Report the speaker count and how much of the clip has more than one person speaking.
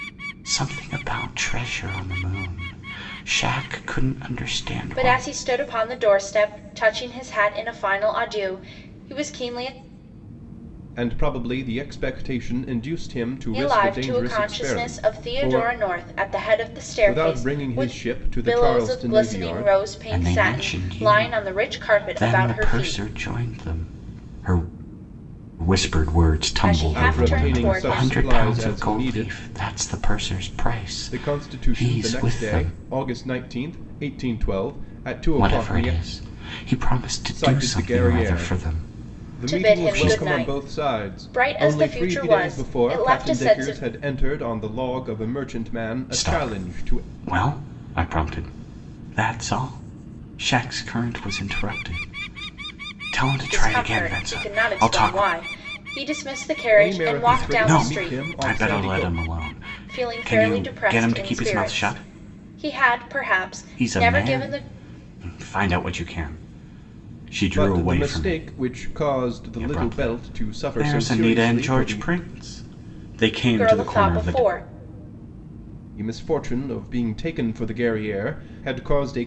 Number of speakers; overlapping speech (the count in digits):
3, about 41%